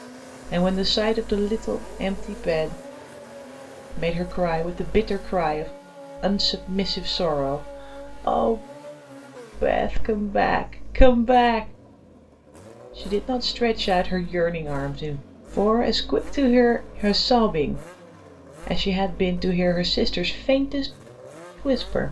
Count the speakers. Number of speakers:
1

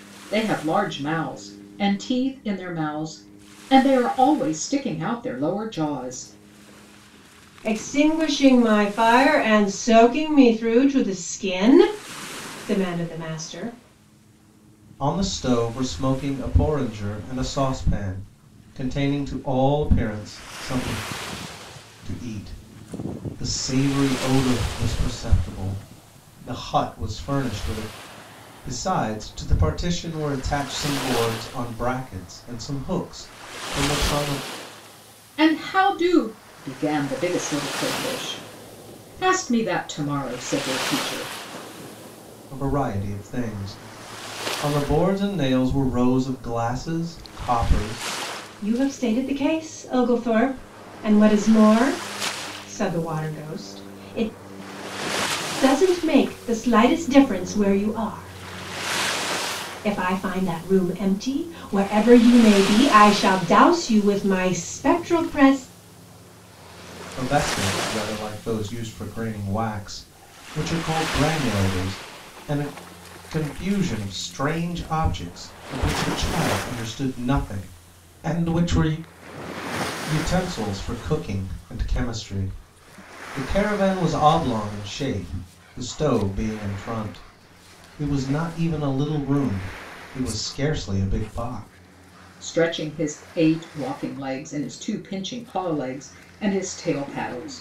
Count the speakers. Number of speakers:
3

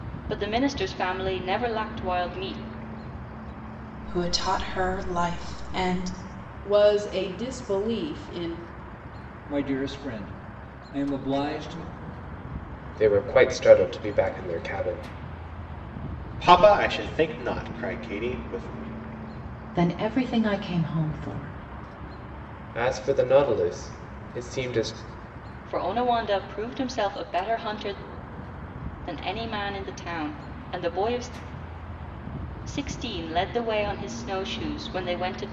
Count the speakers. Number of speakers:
7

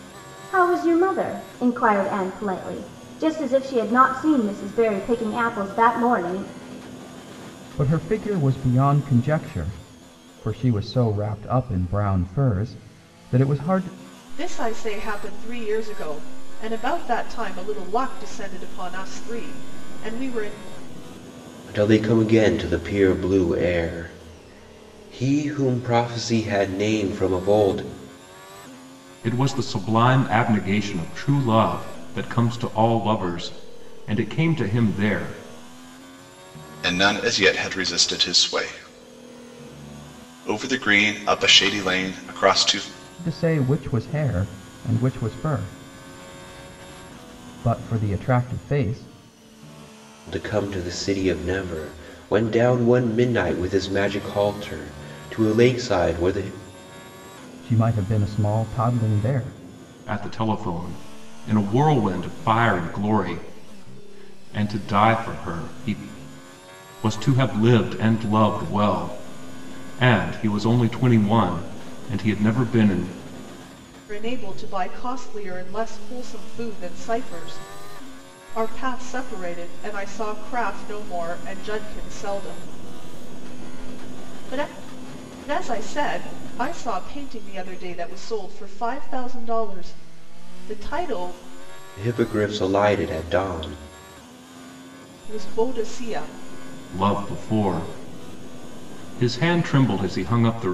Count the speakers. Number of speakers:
6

